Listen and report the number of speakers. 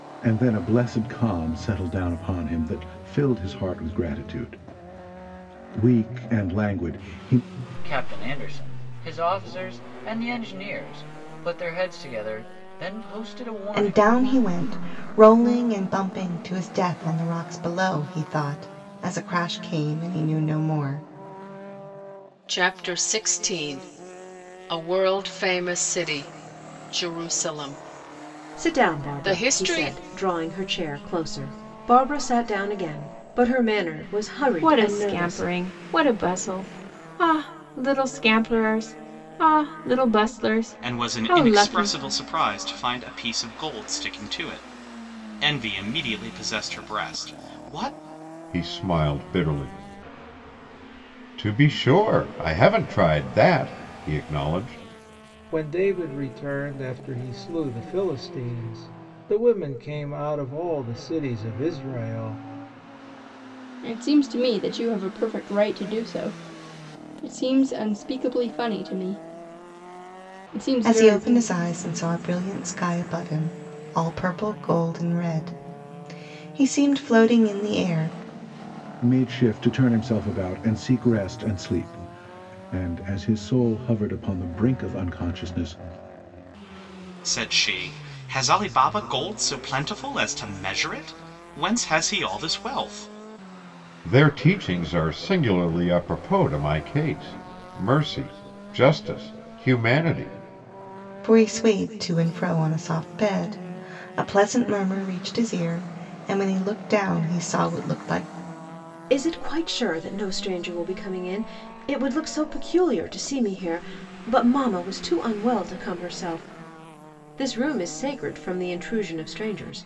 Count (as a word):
ten